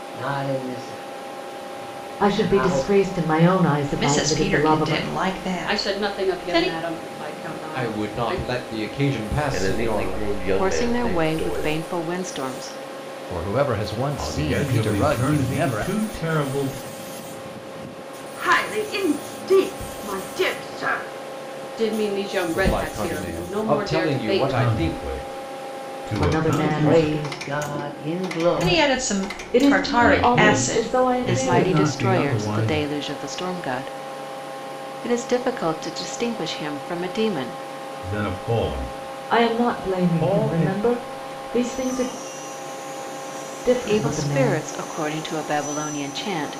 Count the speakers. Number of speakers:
10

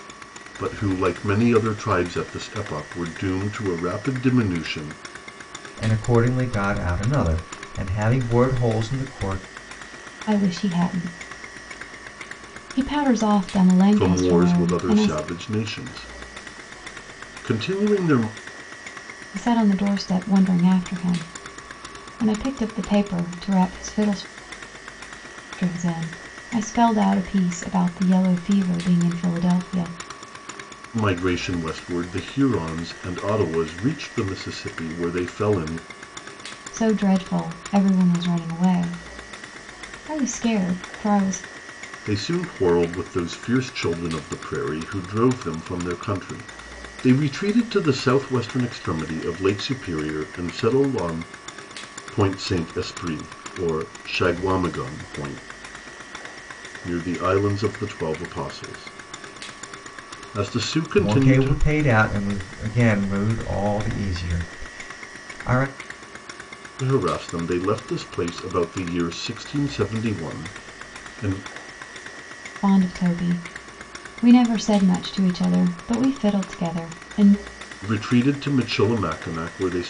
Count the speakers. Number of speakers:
3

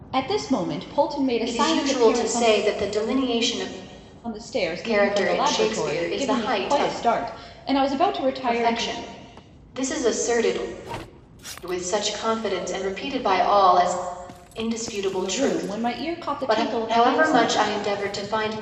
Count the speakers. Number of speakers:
2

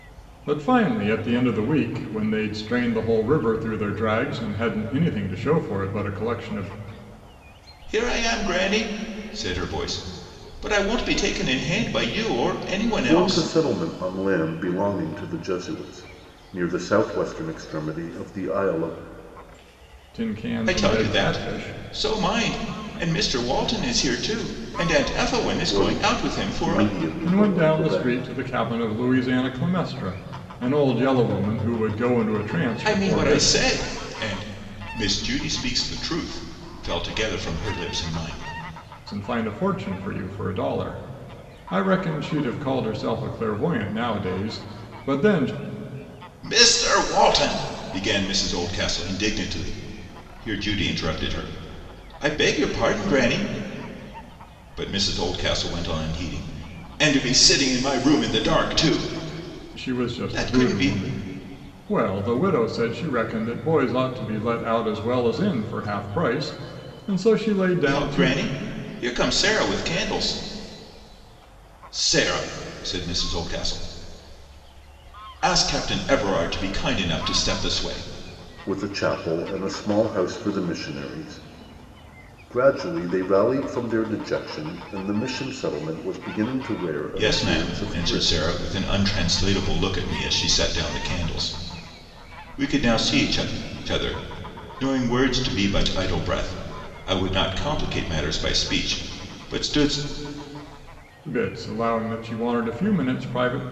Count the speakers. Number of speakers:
3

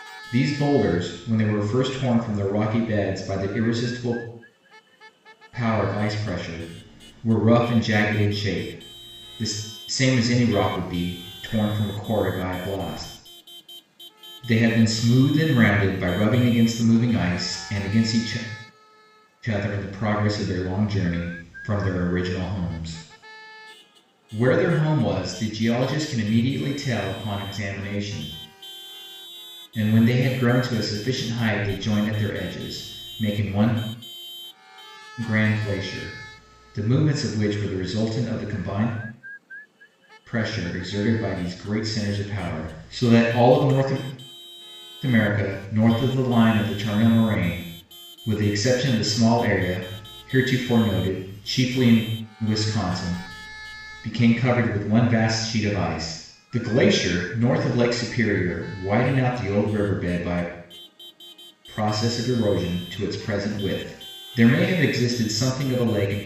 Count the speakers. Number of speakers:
1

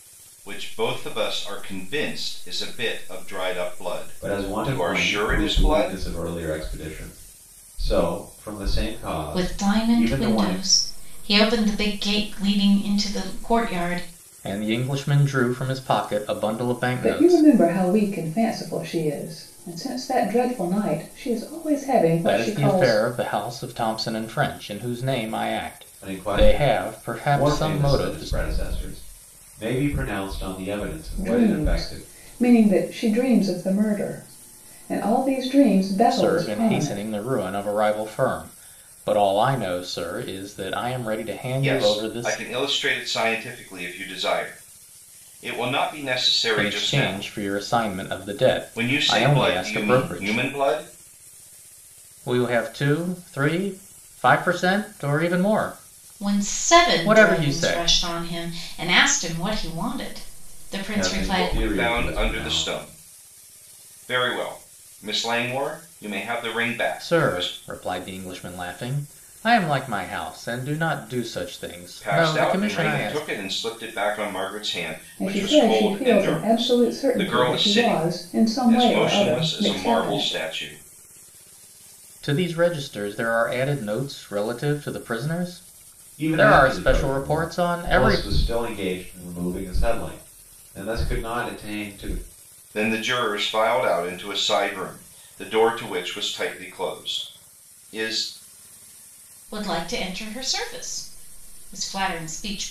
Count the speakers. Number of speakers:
5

